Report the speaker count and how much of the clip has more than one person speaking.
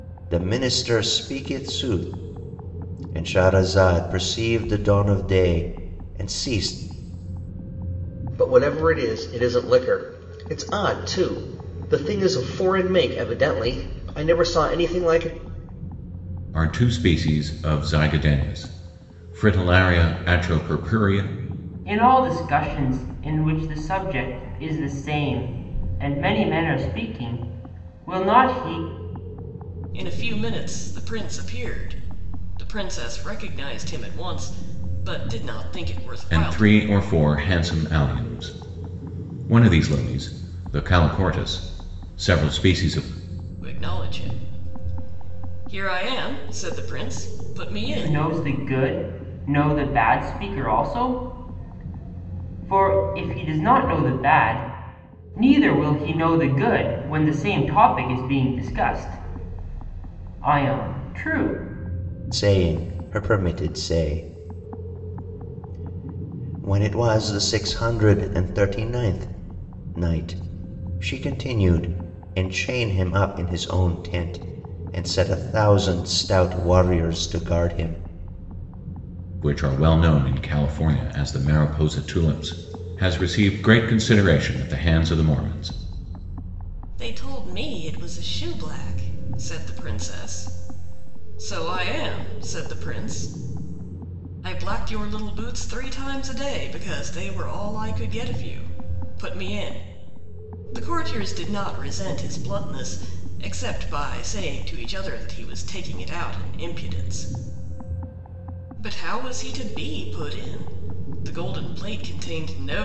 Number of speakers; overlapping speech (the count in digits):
5, about 1%